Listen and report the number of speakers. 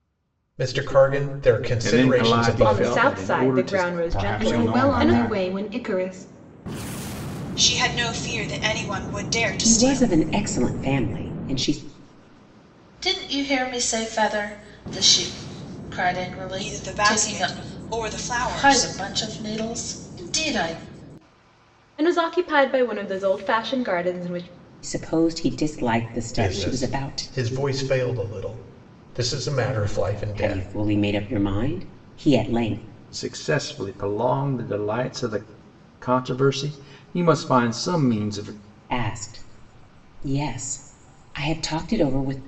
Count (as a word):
eight